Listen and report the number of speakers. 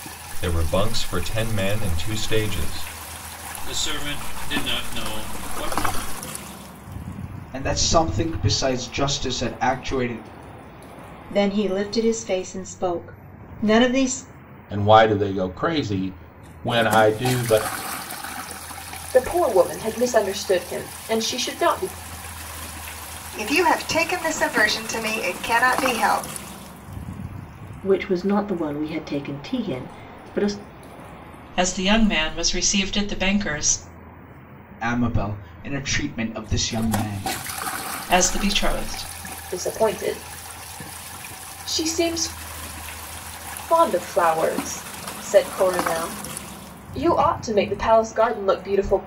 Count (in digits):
9